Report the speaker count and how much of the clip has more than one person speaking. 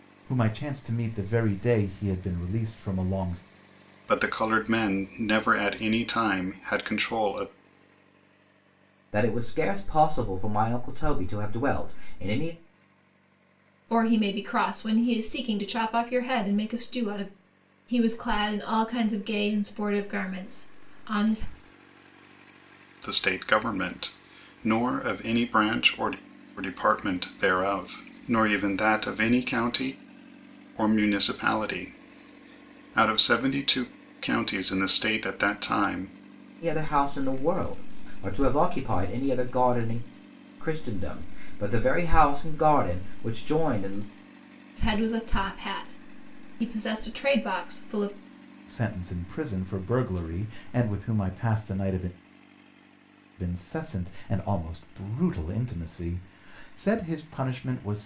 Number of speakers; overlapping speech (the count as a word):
four, no overlap